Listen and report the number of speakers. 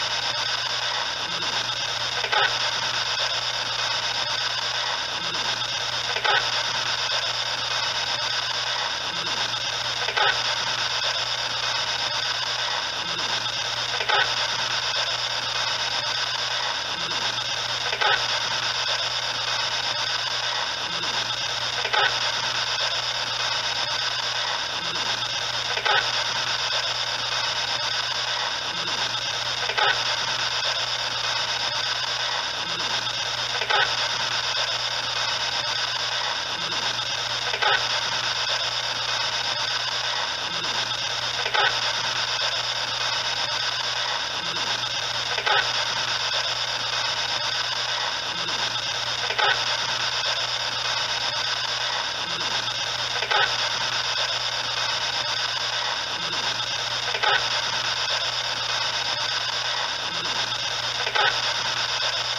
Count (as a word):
zero